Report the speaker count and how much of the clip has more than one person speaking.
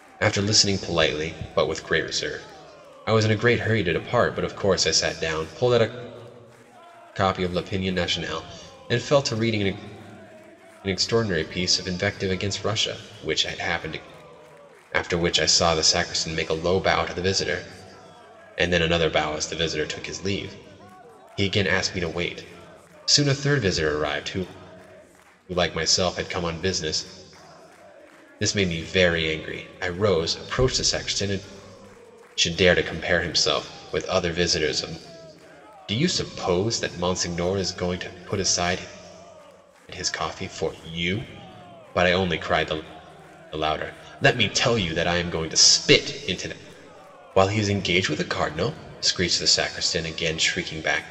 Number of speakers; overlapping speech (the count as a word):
one, no overlap